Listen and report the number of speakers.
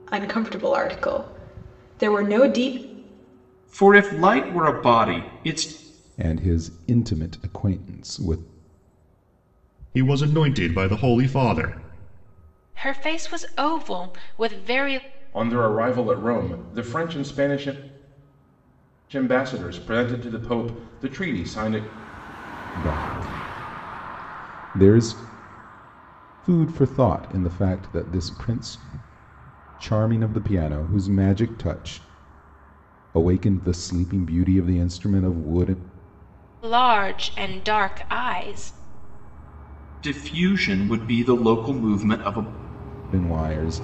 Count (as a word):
six